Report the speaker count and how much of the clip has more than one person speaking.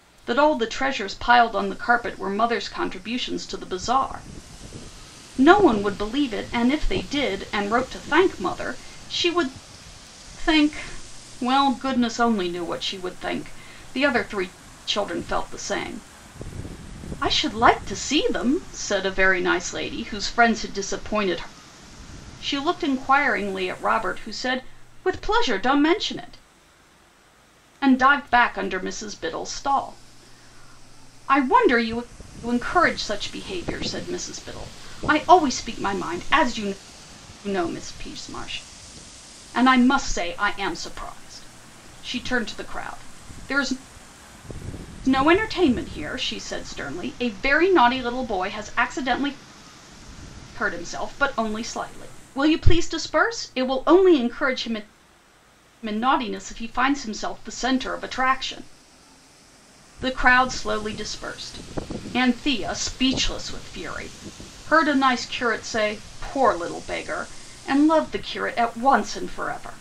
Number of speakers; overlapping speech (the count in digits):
1, no overlap